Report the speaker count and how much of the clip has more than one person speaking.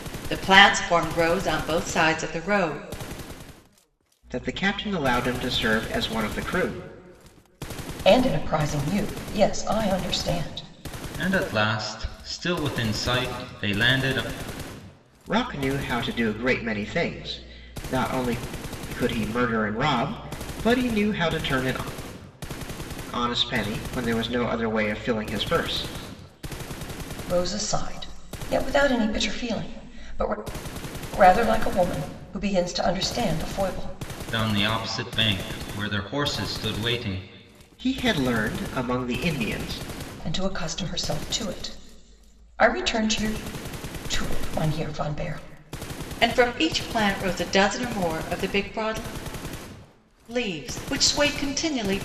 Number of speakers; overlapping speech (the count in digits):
4, no overlap